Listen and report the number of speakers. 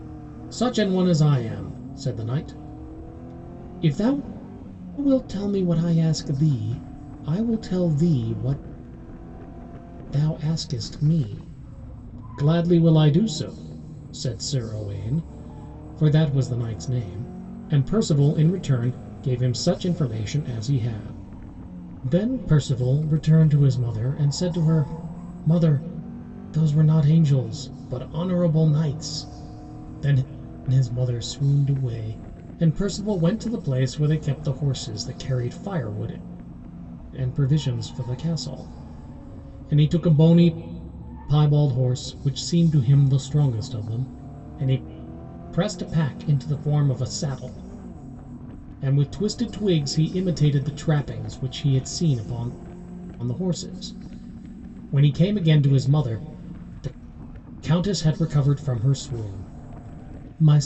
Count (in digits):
1